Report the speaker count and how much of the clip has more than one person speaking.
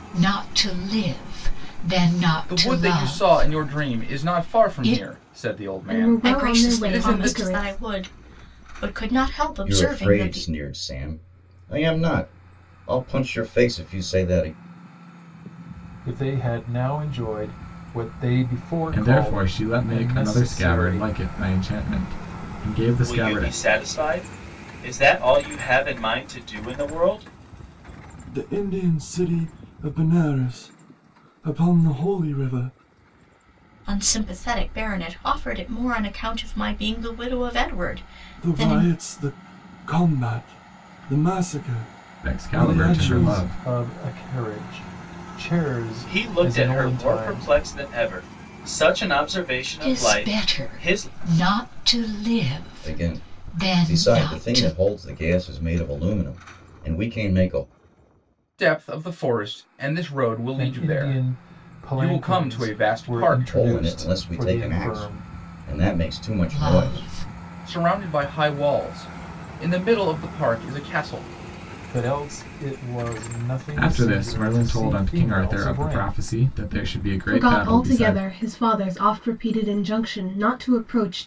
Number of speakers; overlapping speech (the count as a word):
nine, about 29%